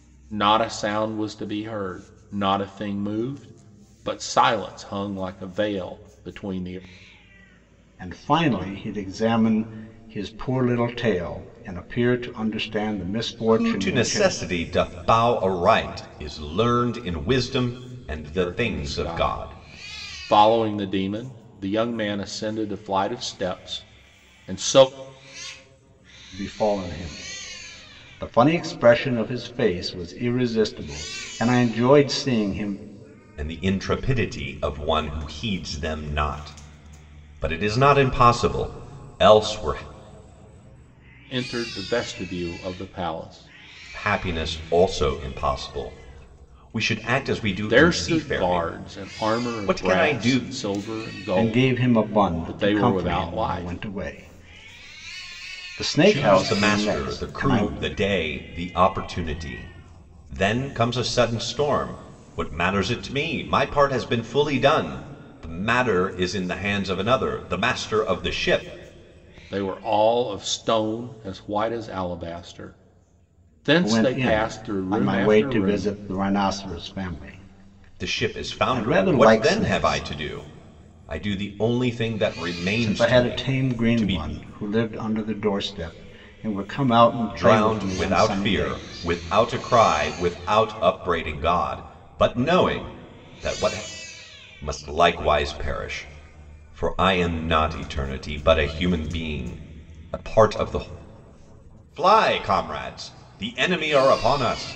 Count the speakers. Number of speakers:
3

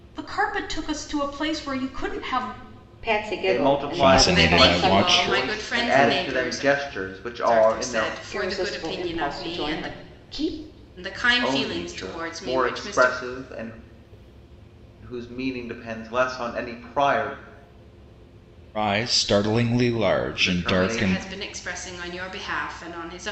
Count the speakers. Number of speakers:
5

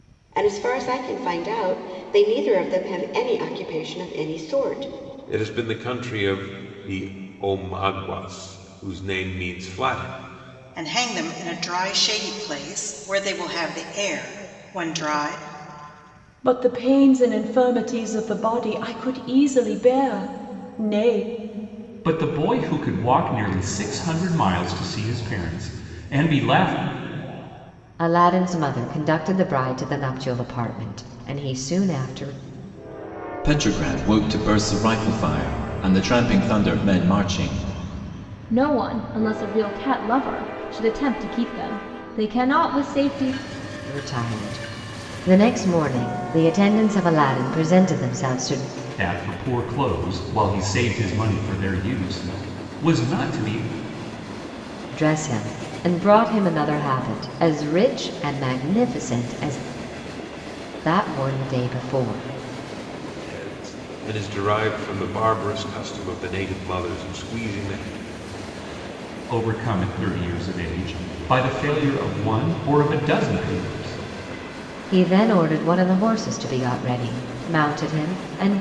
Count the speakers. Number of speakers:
8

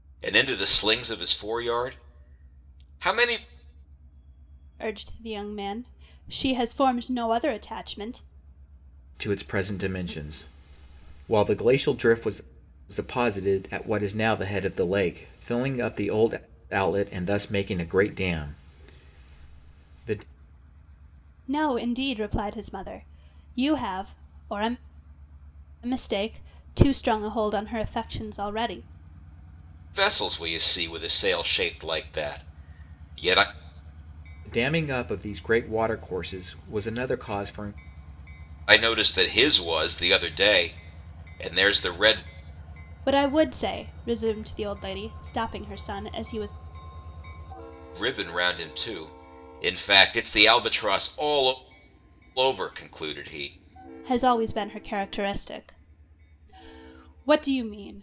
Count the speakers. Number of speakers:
3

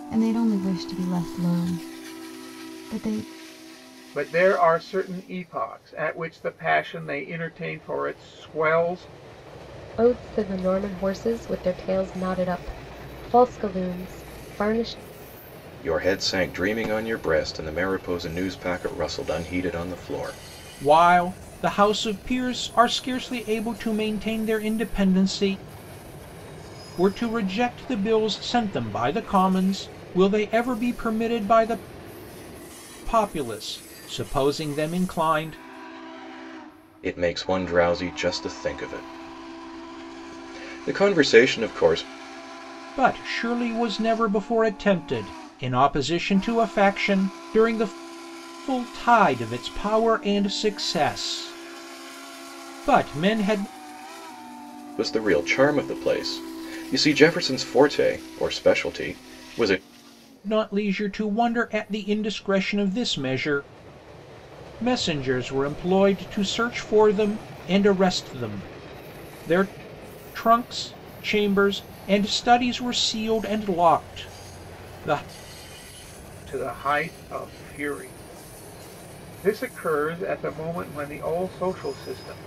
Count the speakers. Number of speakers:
5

